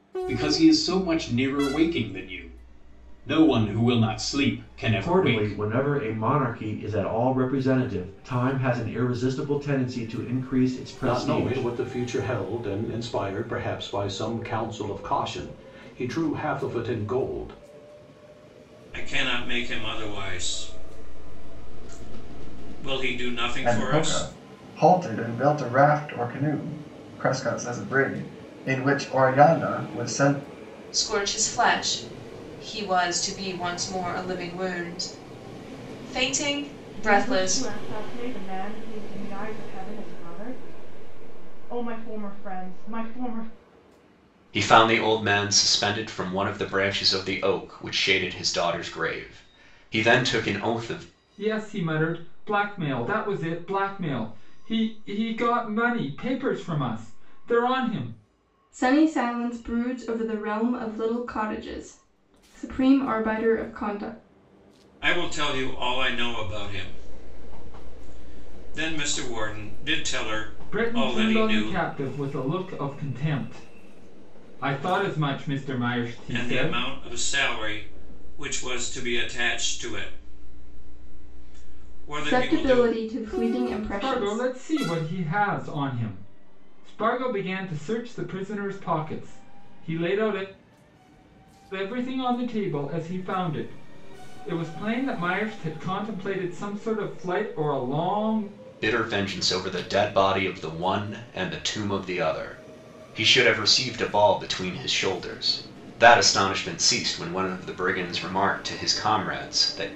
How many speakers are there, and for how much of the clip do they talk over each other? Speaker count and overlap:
10, about 5%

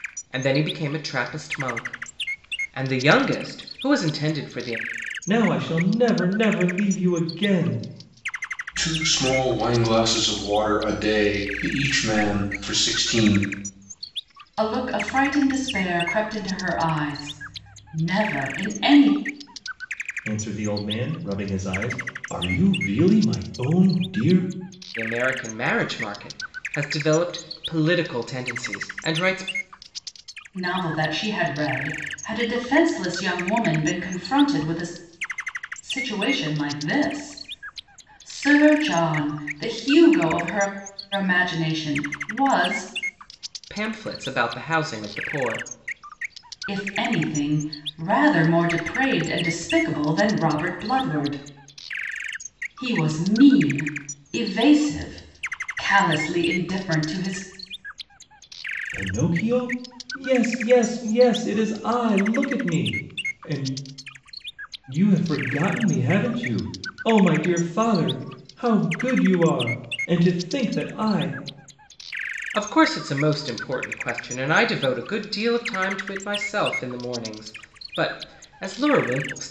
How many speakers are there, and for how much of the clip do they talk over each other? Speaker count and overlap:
4, no overlap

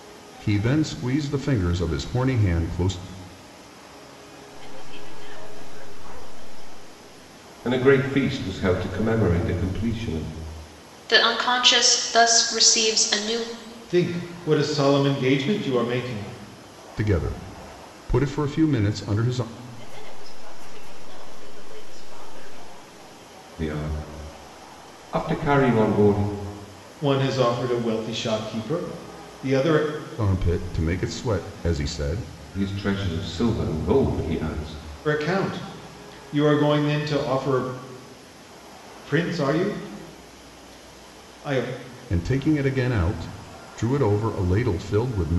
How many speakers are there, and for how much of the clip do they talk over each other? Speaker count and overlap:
5, no overlap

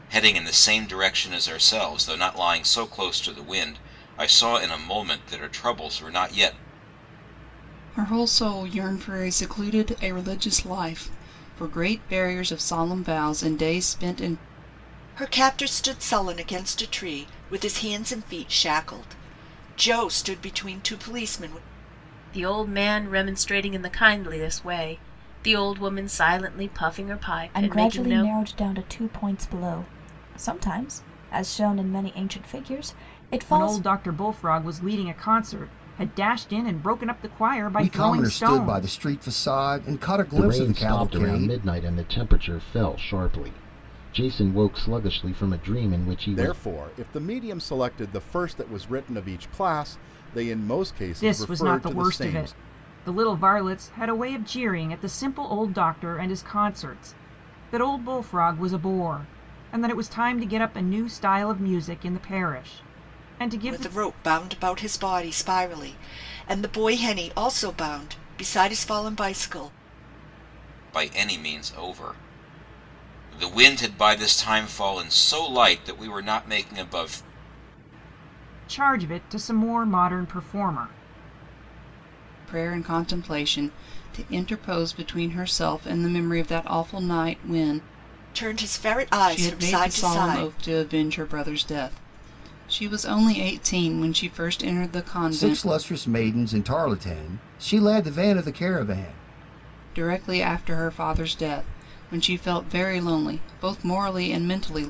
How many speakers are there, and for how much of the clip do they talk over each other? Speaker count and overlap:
9, about 7%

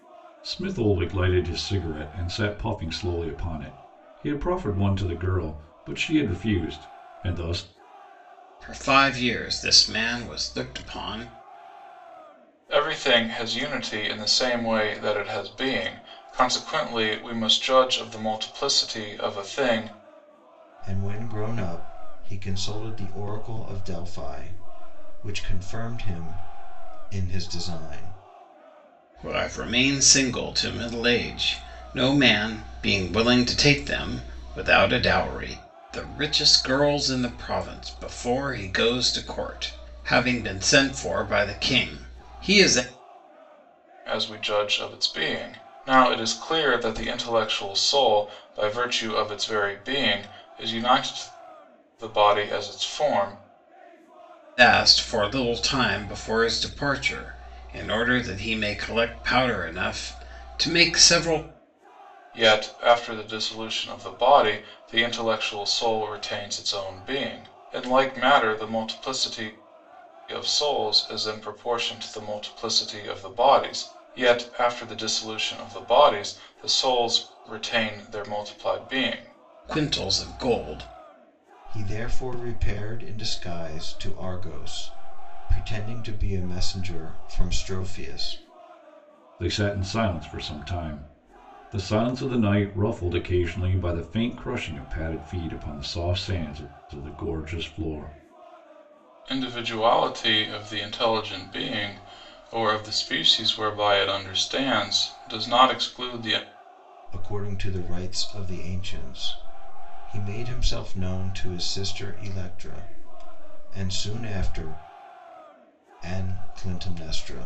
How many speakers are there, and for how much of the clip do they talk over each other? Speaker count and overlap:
4, no overlap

